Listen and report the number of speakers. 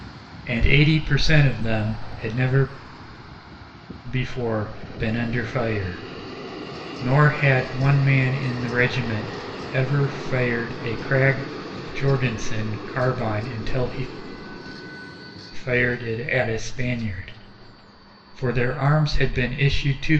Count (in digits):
1